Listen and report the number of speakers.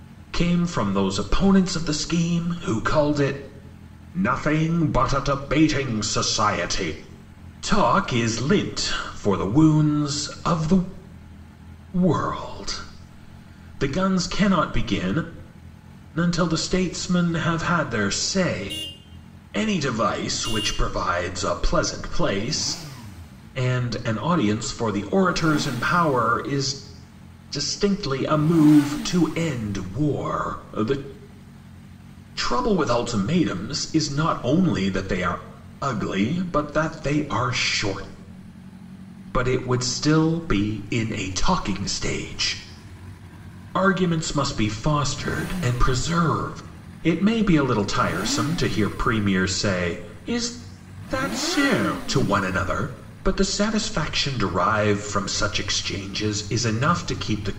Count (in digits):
1